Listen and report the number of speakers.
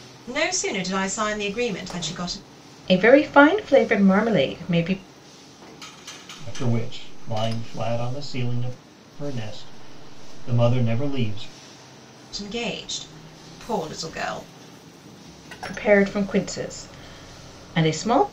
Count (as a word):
three